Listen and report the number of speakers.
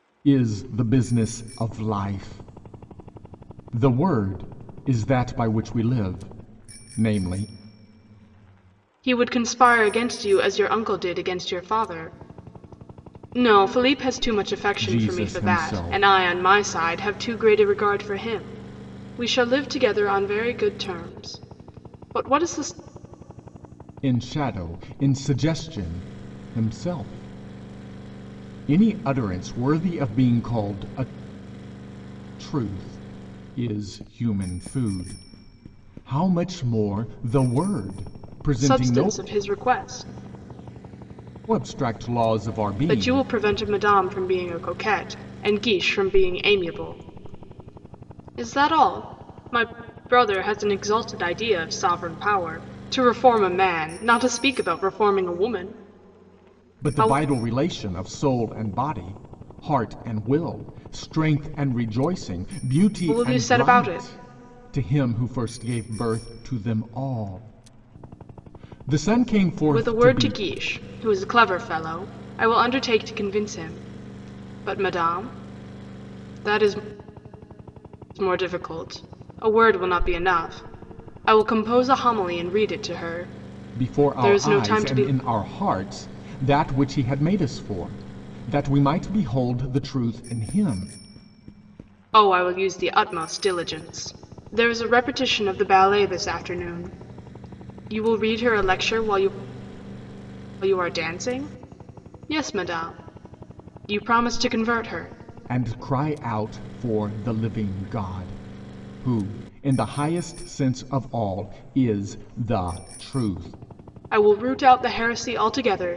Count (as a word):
two